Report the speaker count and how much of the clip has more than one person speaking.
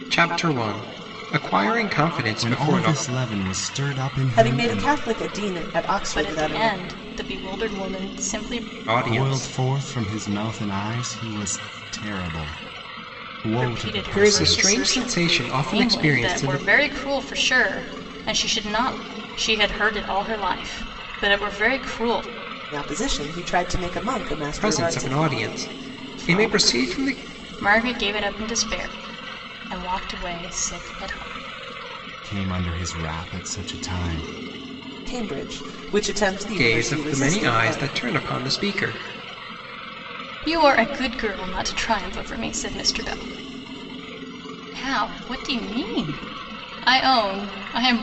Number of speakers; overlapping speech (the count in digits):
4, about 18%